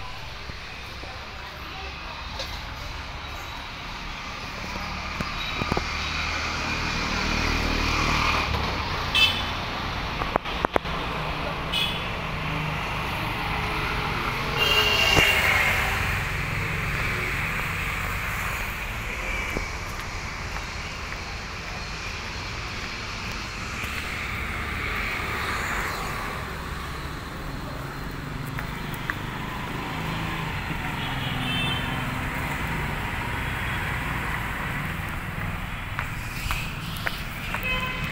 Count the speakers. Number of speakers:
0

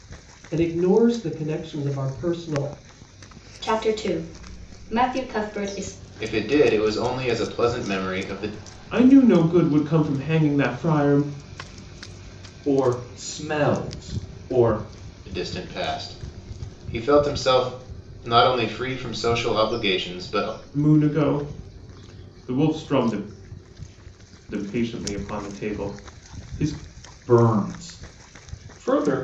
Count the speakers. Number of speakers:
5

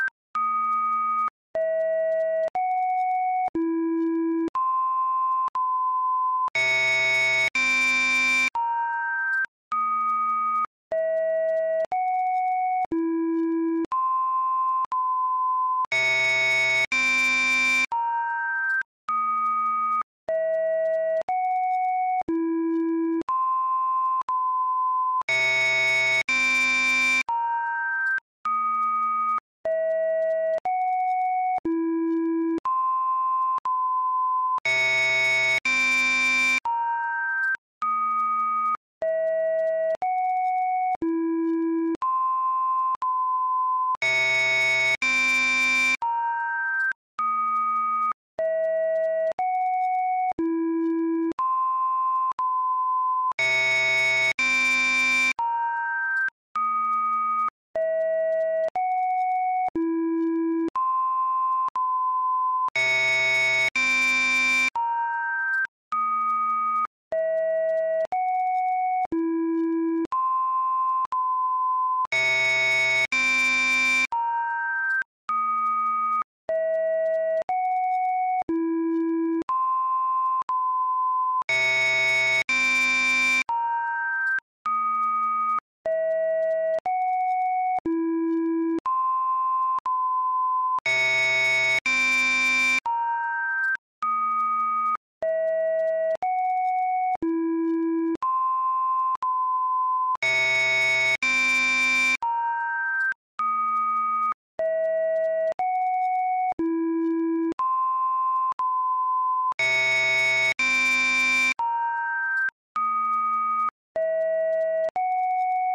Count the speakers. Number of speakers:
0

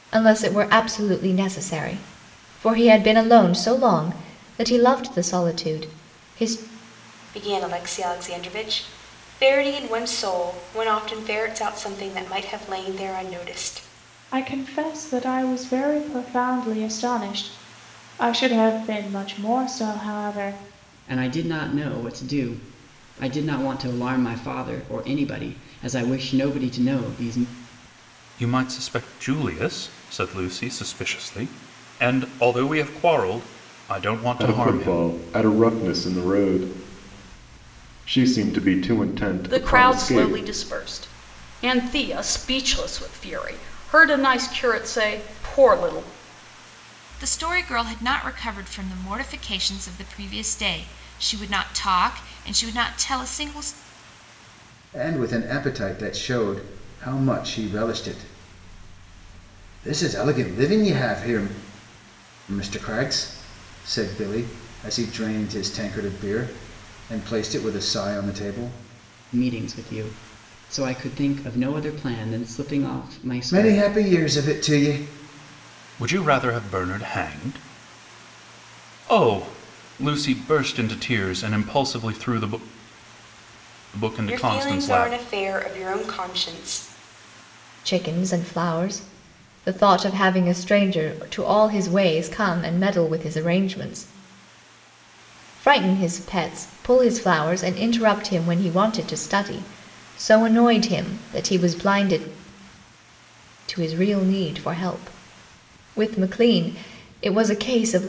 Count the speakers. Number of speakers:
9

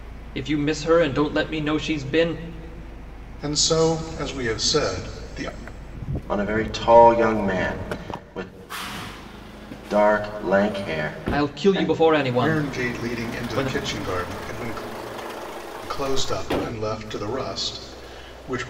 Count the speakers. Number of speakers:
3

